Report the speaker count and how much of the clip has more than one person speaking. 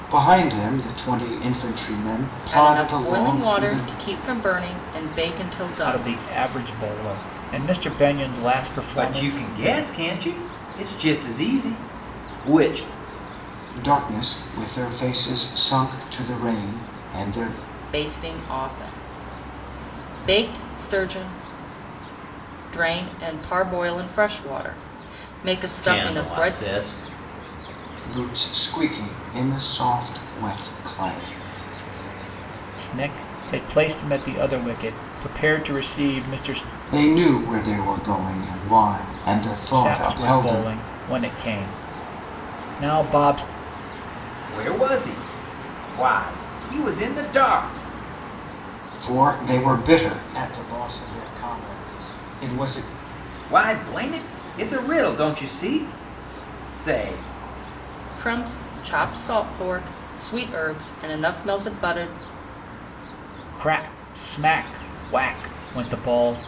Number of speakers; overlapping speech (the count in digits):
4, about 7%